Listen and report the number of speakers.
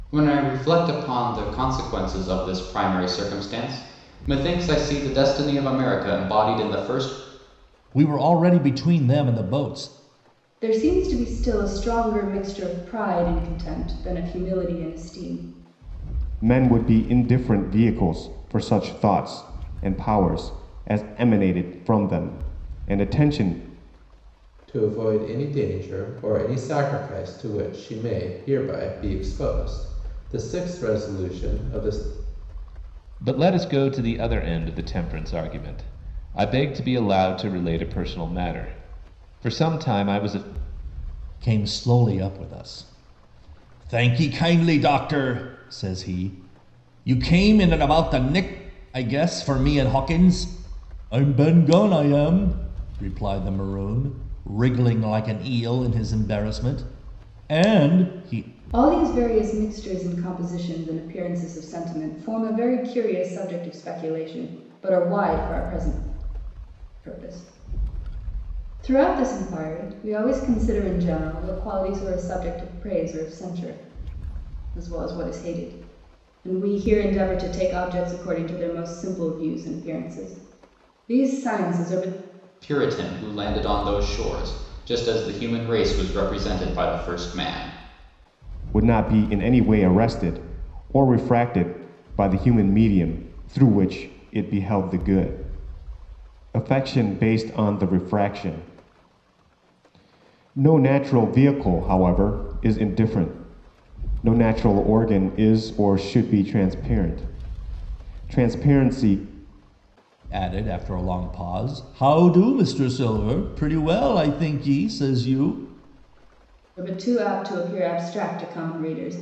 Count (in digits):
6